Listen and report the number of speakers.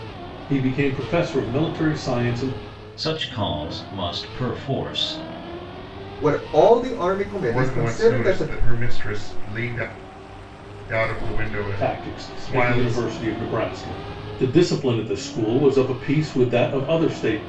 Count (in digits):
4